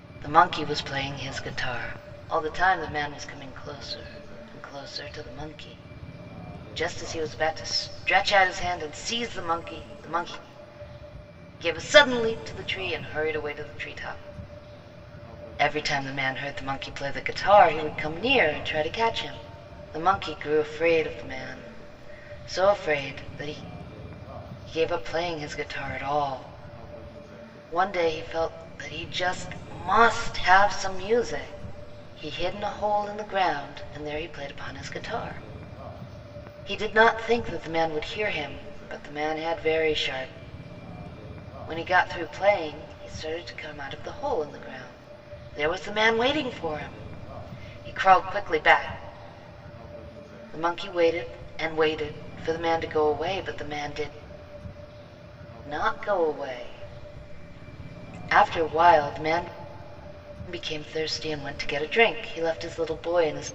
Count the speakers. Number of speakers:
one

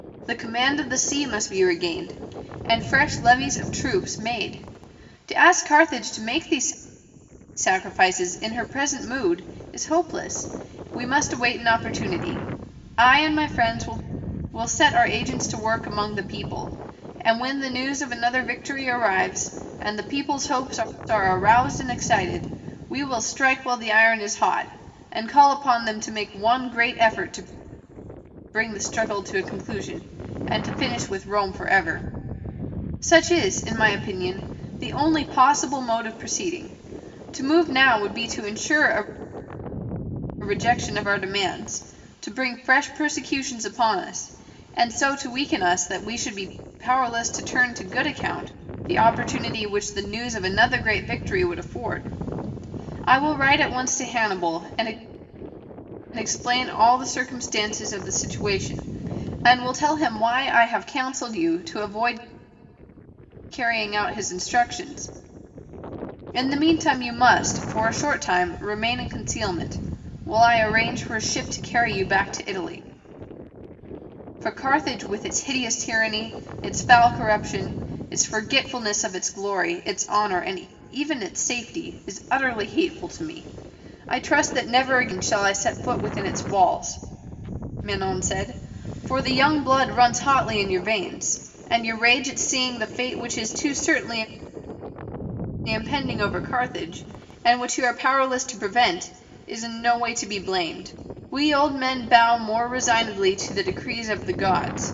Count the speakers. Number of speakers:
one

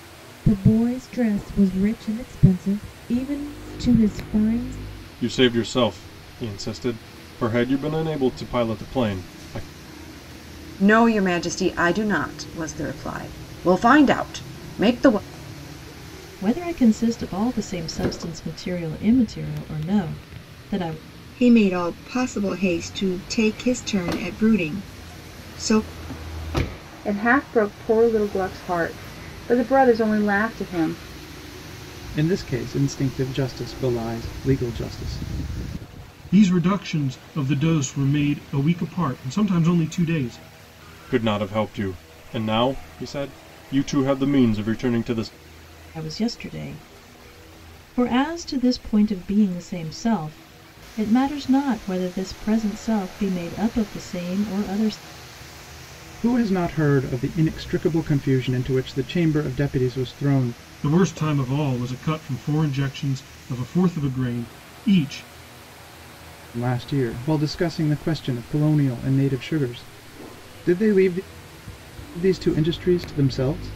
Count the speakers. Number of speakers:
eight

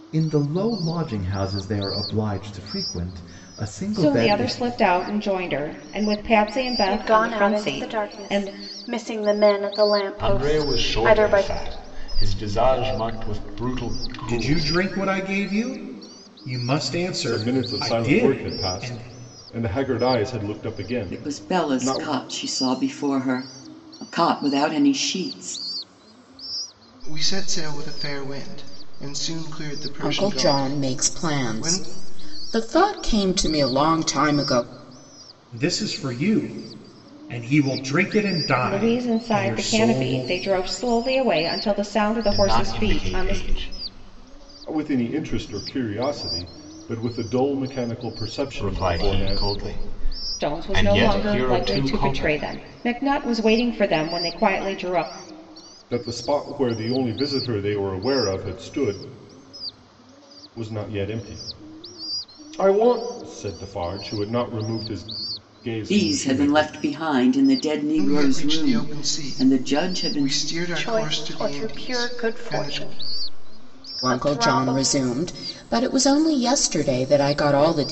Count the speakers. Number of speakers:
nine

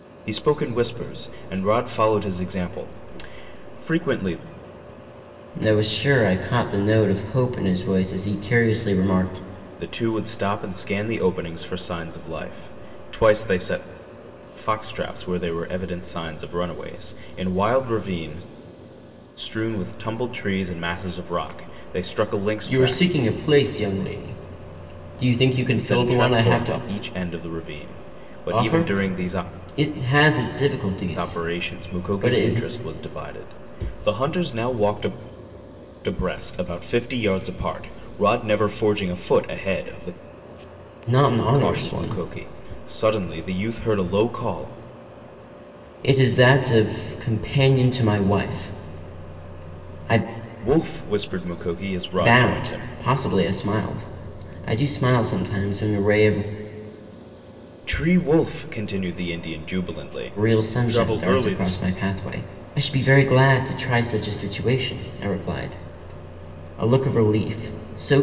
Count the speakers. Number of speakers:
two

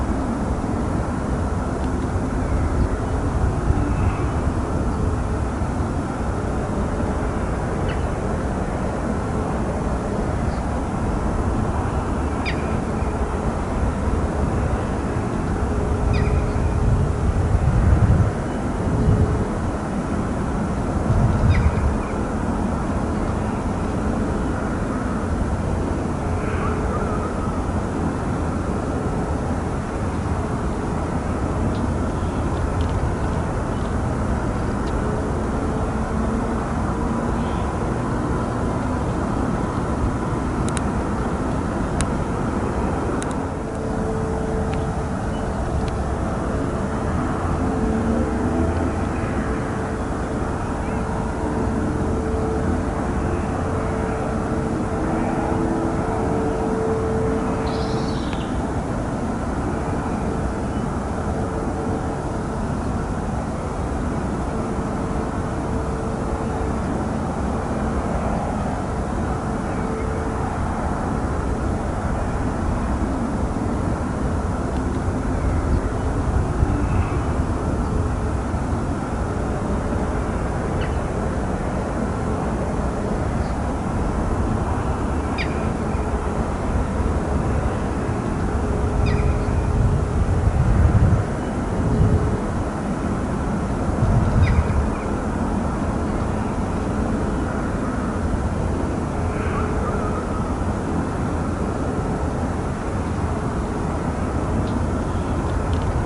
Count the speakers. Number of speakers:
zero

